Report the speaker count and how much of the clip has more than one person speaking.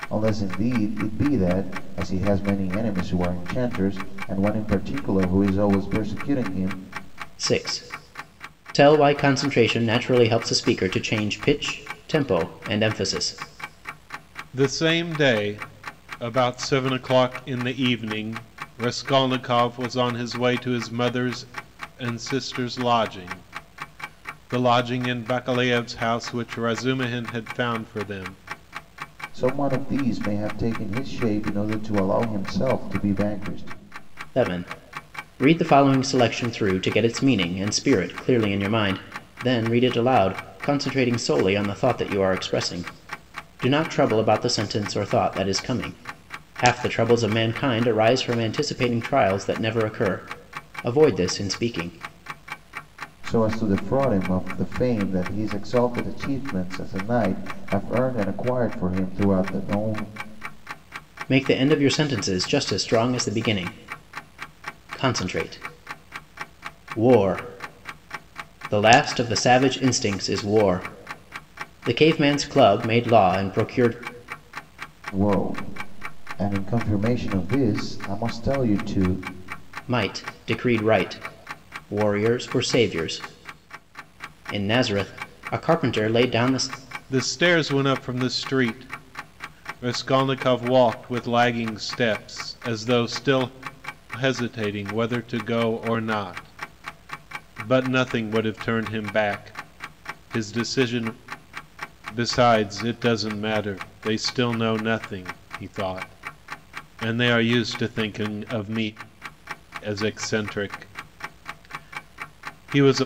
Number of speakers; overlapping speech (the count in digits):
3, no overlap